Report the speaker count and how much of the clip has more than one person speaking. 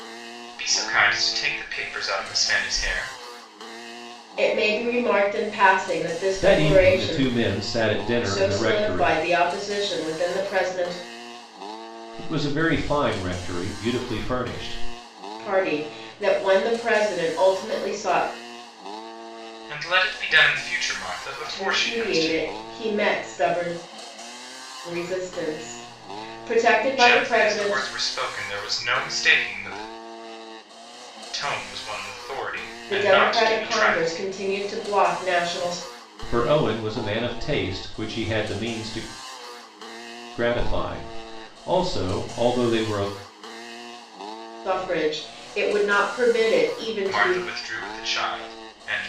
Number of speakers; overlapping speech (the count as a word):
three, about 11%